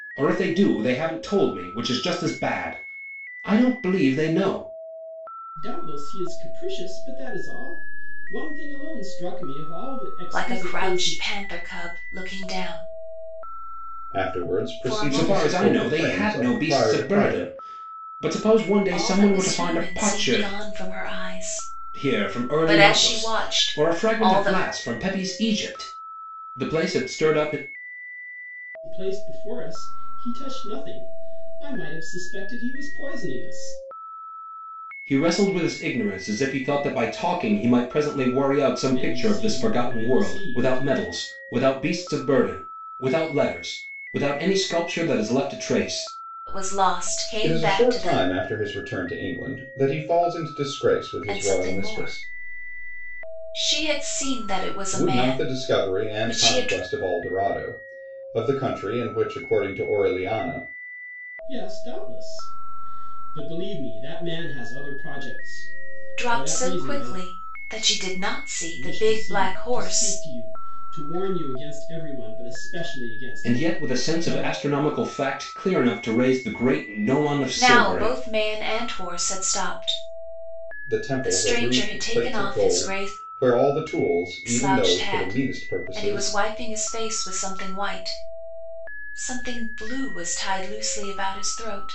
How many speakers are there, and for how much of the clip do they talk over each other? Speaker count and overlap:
4, about 25%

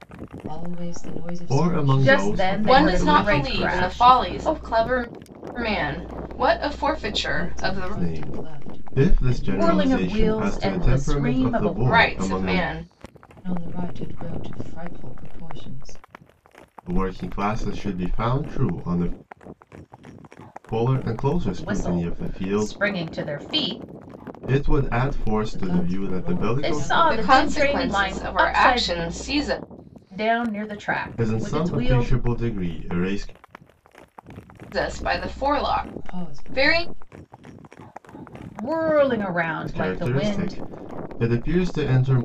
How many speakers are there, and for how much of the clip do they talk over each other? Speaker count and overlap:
4, about 38%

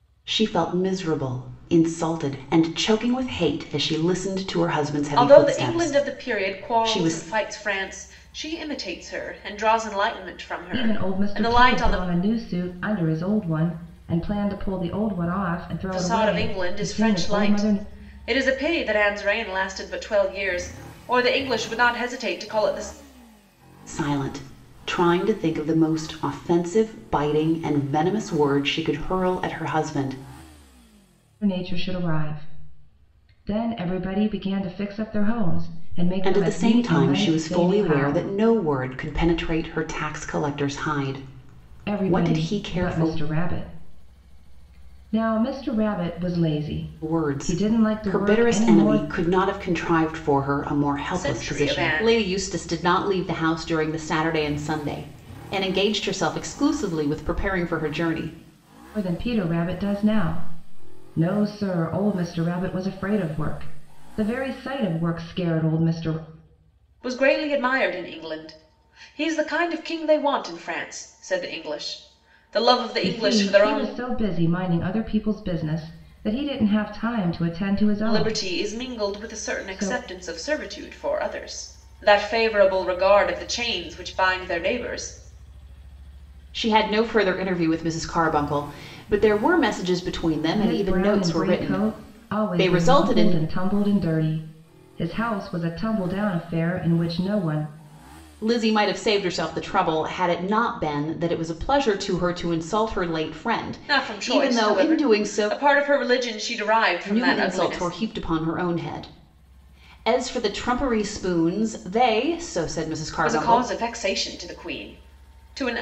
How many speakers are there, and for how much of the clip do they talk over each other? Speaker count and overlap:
3, about 18%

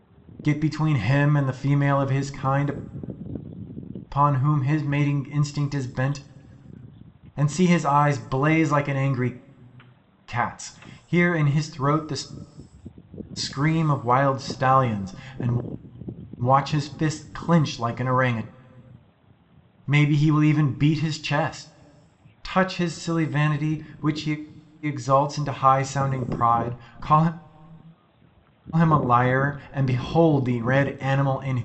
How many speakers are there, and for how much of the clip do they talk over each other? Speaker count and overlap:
1, no overlap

